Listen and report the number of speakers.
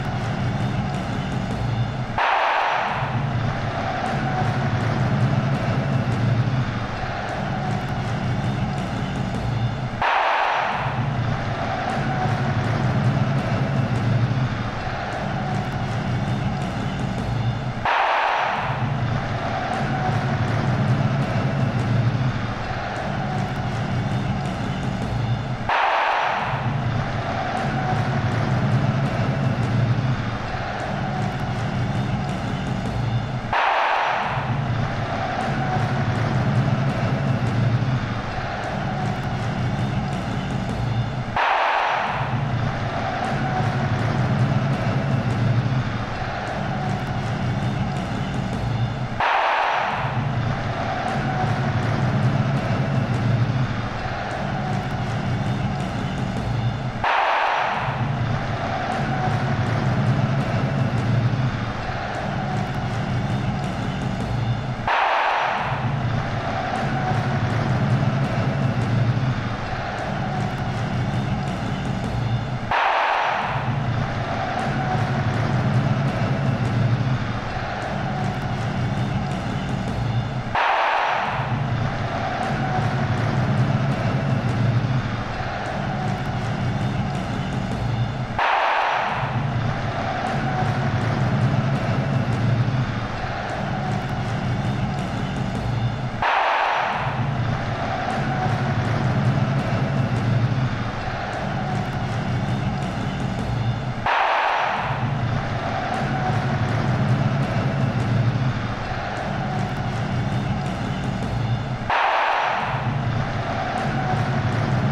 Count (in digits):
0